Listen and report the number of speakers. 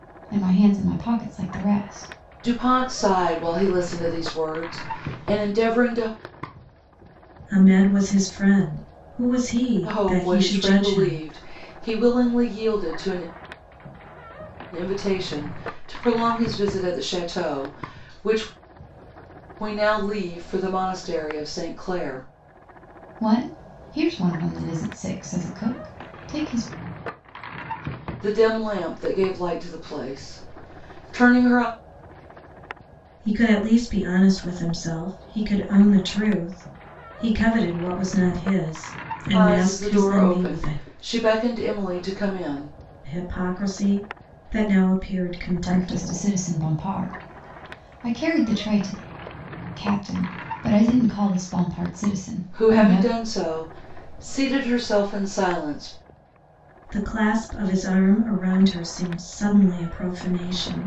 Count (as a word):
three